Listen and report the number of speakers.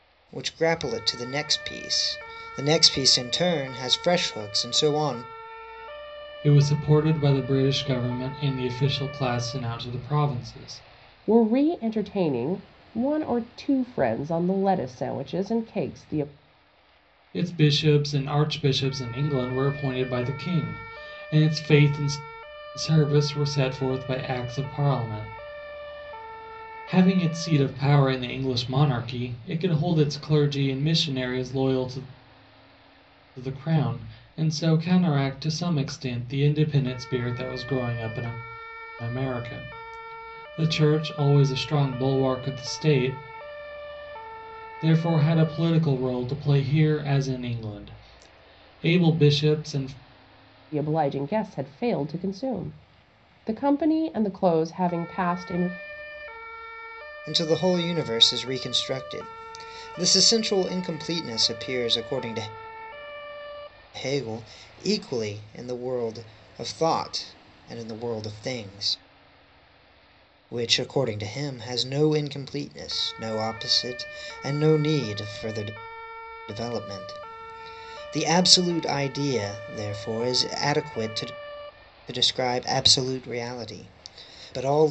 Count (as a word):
three